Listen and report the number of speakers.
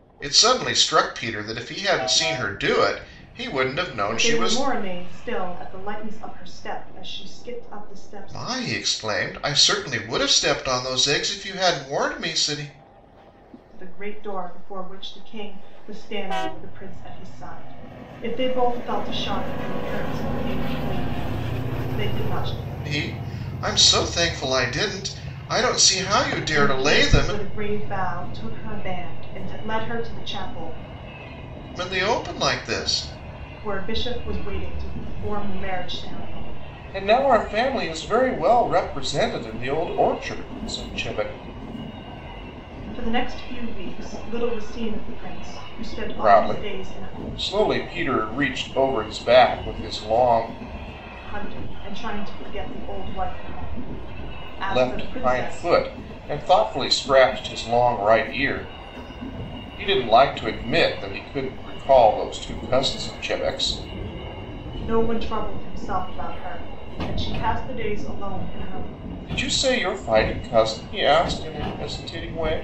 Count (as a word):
two